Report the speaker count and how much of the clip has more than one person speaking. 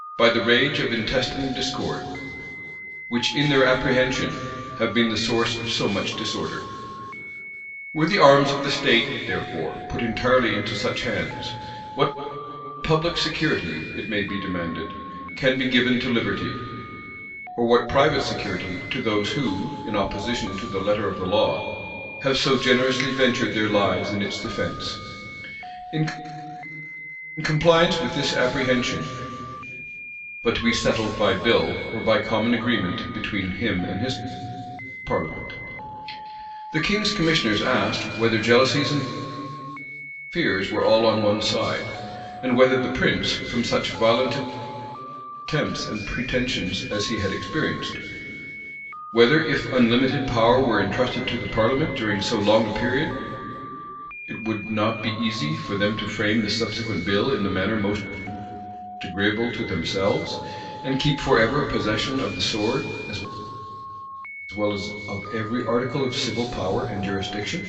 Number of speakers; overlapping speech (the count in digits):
1, no overlap